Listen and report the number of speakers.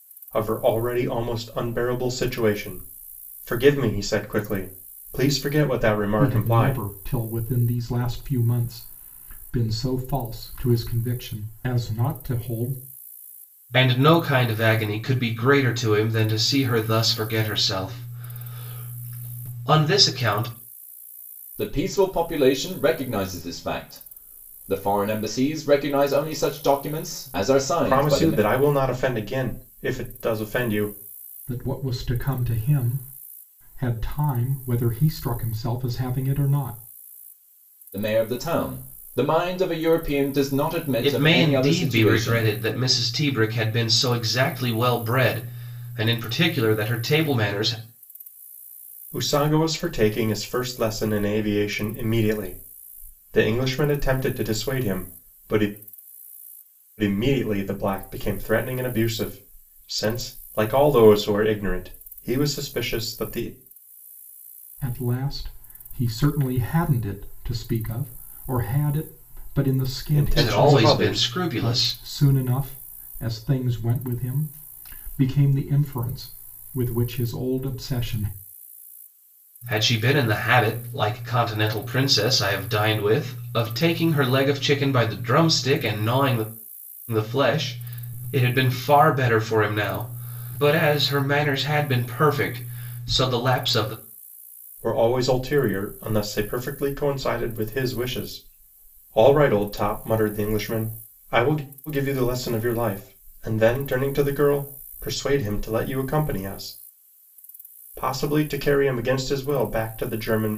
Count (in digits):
4